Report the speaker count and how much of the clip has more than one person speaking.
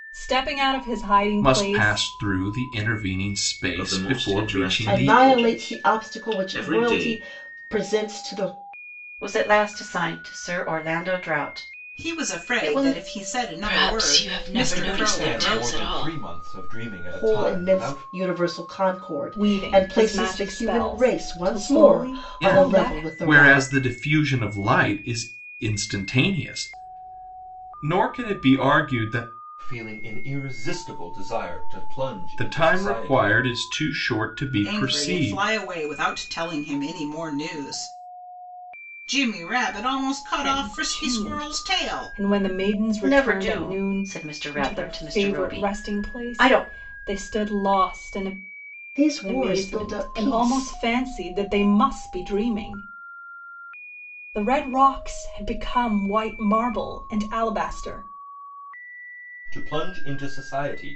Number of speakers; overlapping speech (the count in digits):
8, about 35%